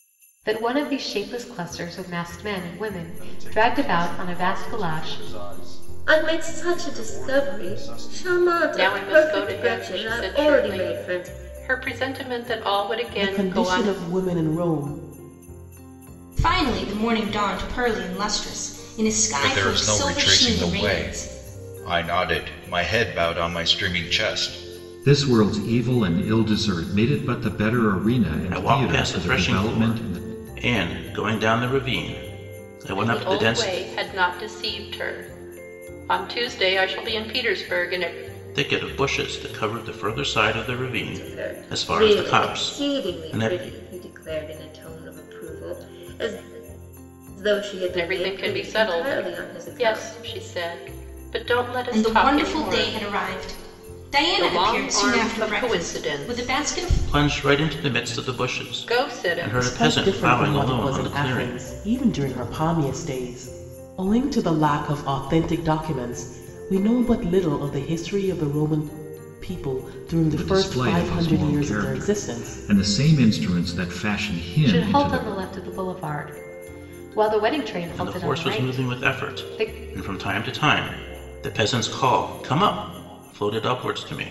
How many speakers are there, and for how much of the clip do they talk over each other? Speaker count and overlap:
nine, about 36%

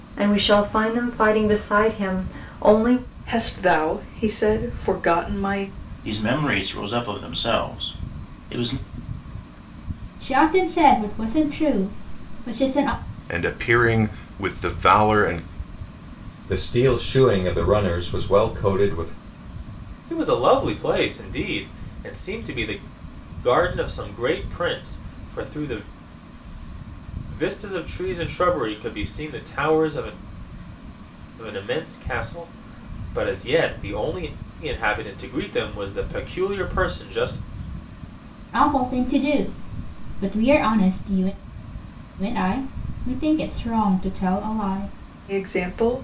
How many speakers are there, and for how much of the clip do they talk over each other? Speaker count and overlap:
seven, no overlap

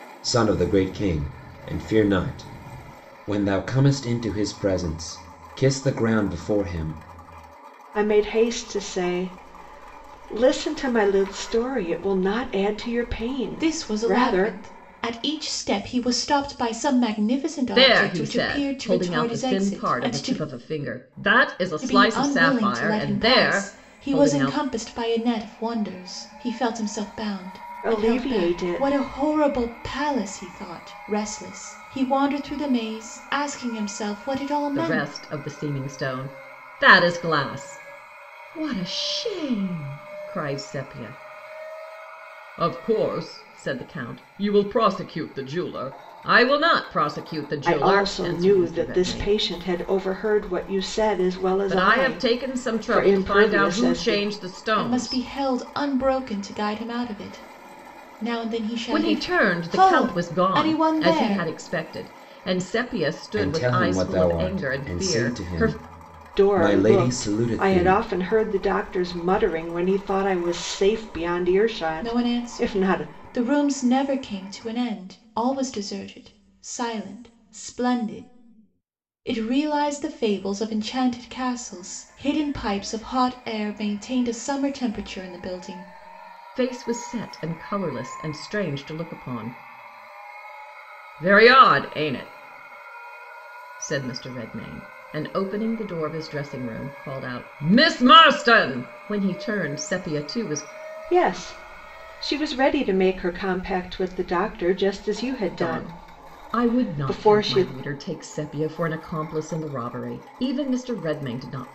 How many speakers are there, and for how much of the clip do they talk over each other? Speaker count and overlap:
four, about 21%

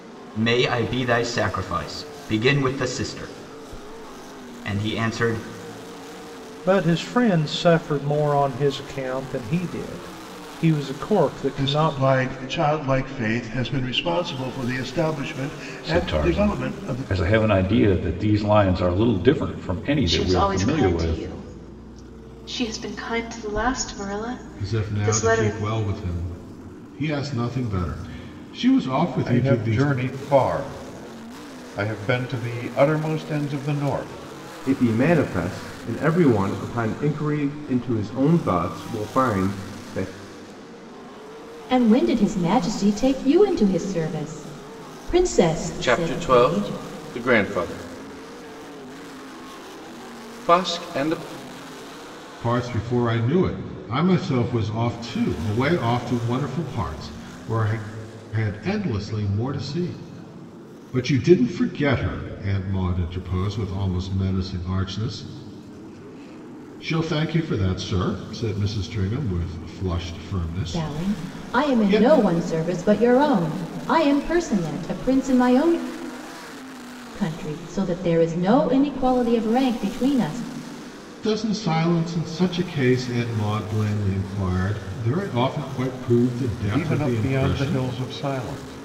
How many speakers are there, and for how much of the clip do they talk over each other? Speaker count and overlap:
ten, about 9%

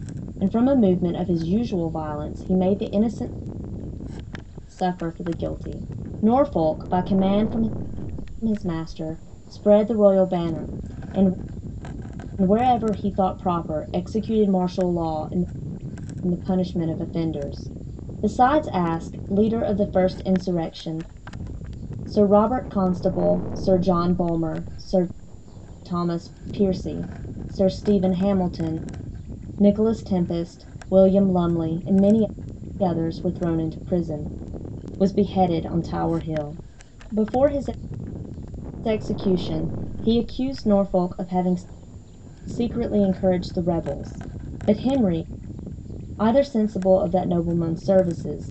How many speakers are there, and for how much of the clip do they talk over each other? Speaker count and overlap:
one, no overlap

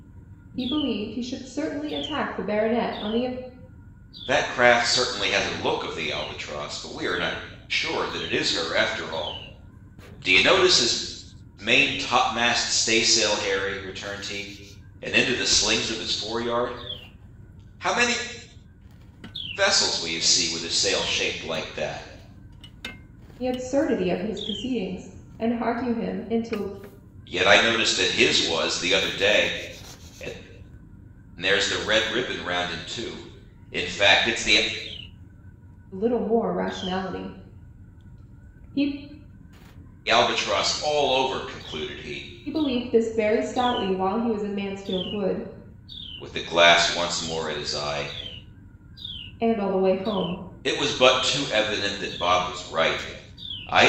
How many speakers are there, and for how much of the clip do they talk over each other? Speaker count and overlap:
two, no overlap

